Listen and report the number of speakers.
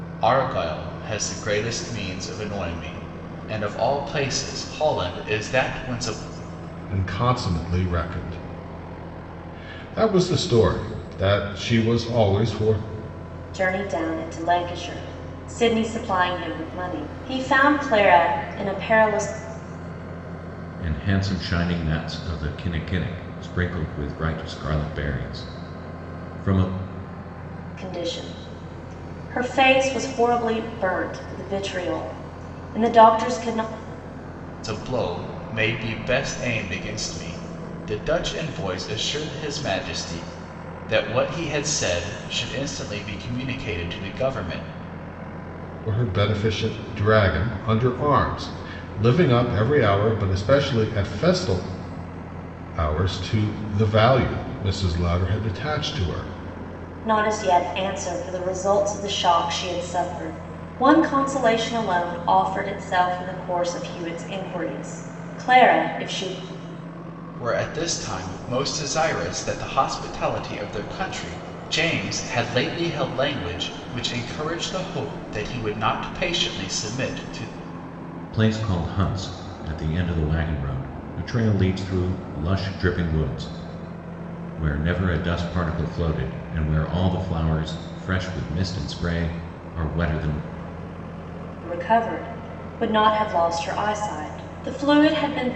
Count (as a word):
four